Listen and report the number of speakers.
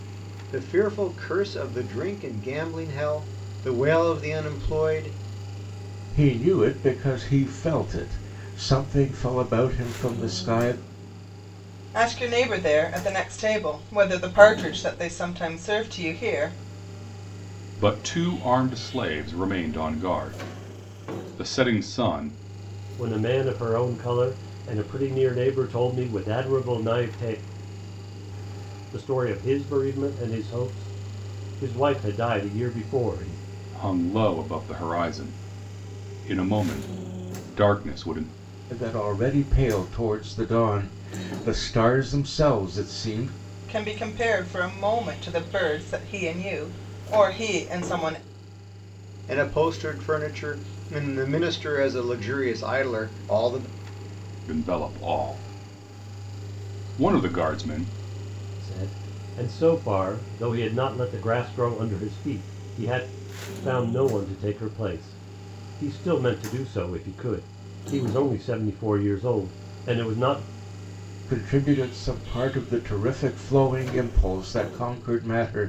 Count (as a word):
five